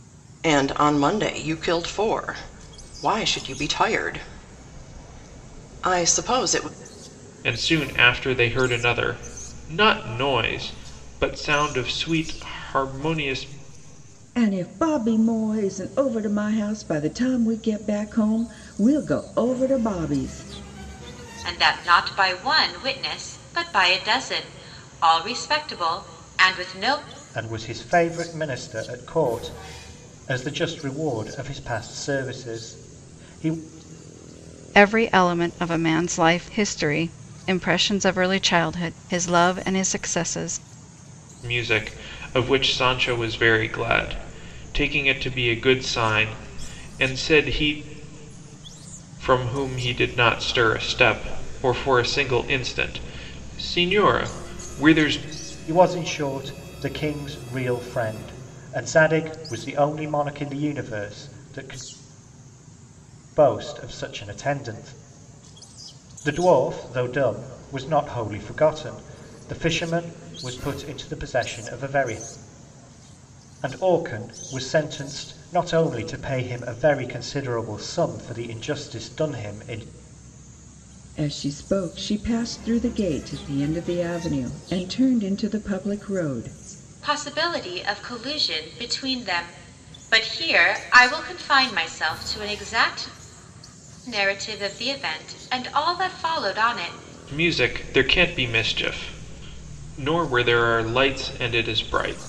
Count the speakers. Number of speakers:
6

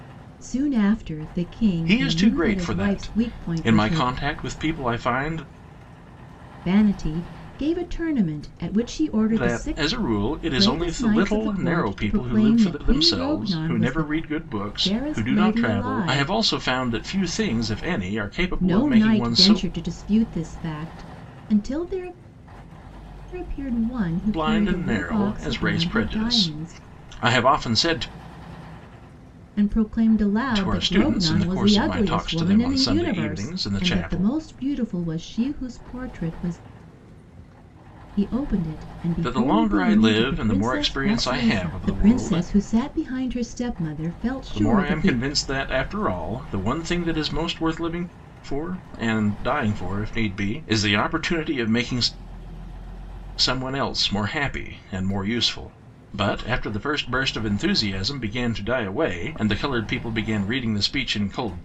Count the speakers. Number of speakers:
2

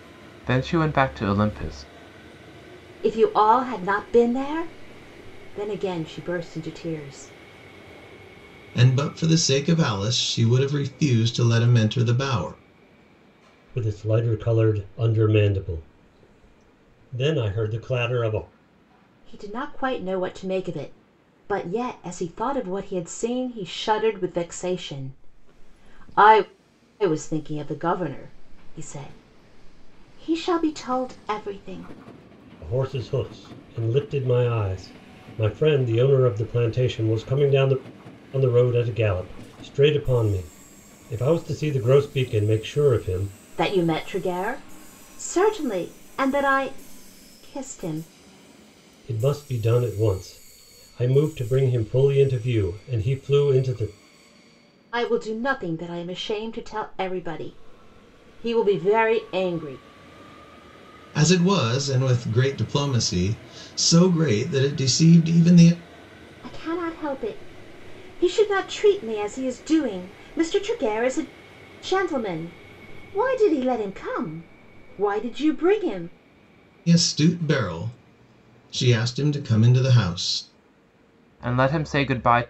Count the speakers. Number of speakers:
4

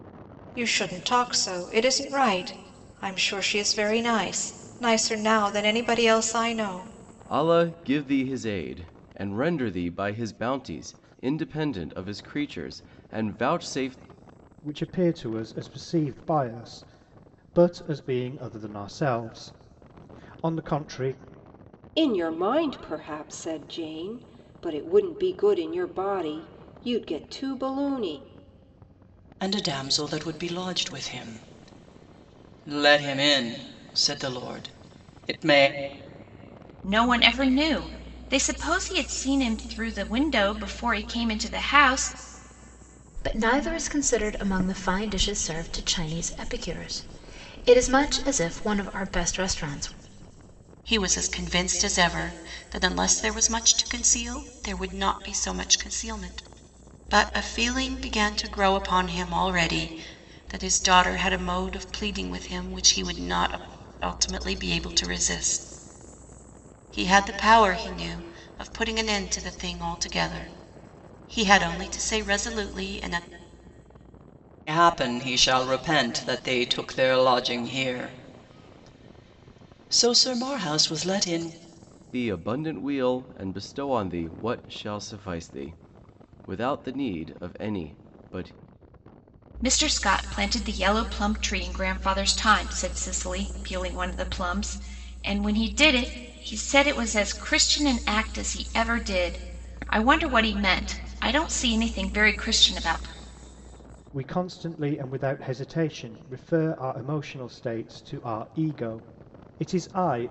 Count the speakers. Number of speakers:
8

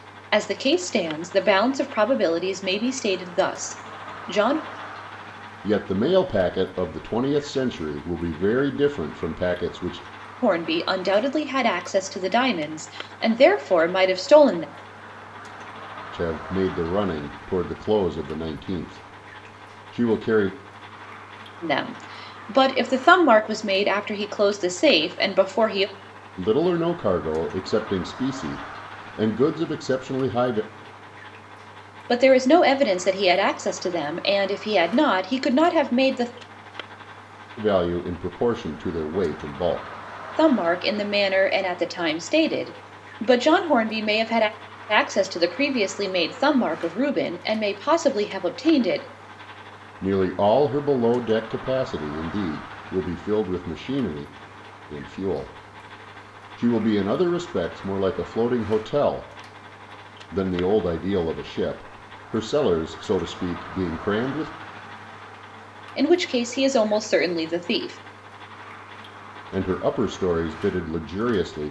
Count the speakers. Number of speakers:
2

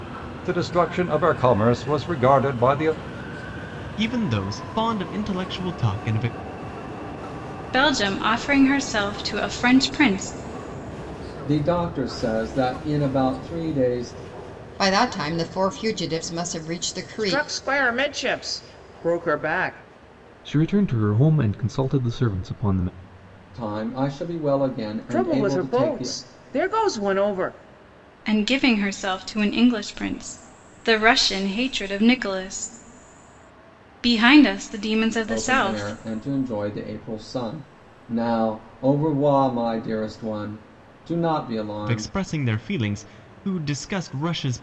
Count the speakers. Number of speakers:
7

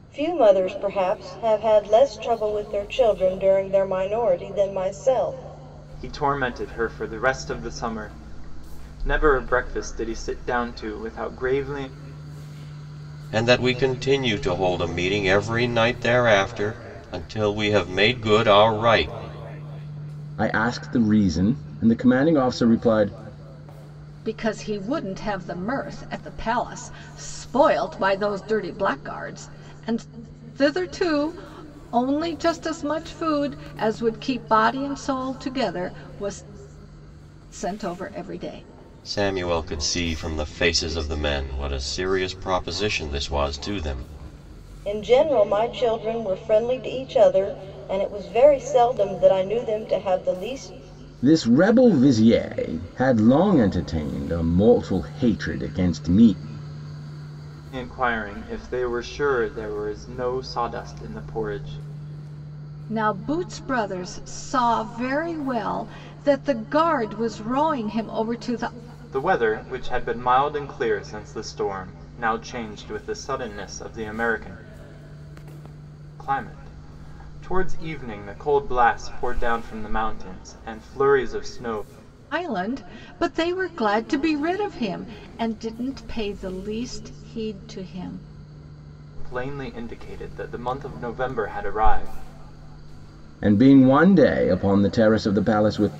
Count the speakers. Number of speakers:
5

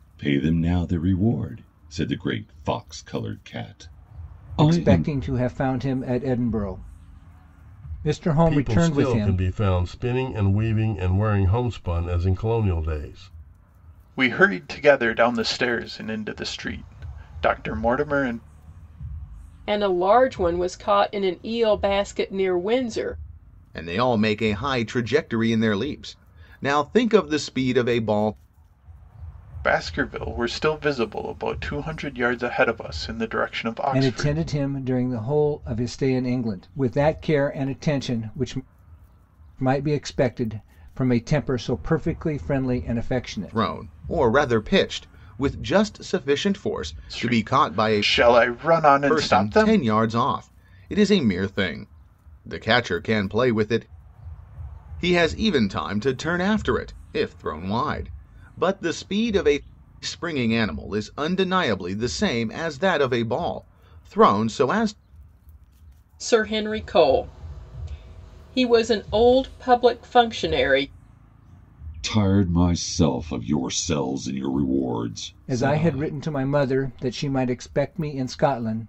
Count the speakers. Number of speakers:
6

